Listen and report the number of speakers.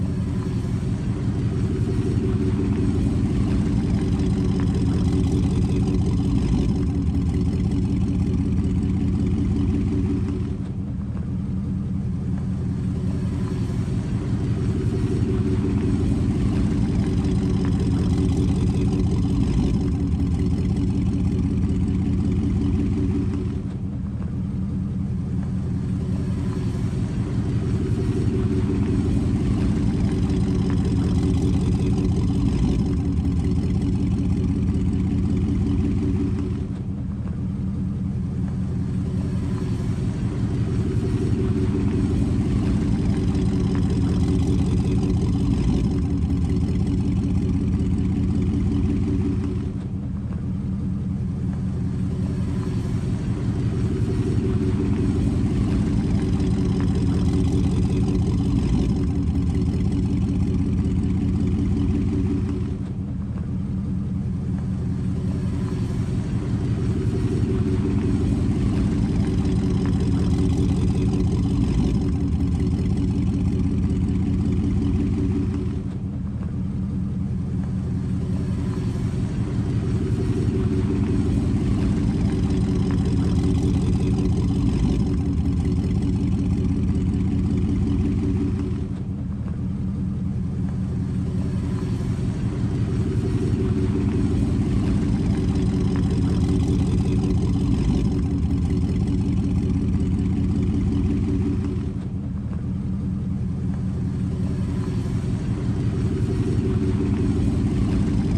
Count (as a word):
zero